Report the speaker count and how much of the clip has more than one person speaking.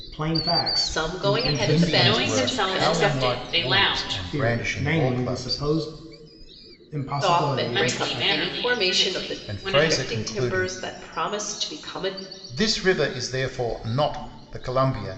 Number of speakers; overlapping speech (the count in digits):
4, about 55%